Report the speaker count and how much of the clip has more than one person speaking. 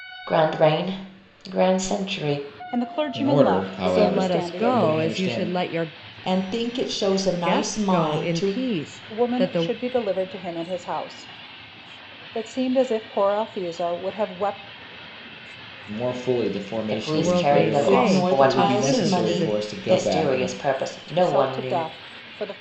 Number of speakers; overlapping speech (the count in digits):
5, about 39%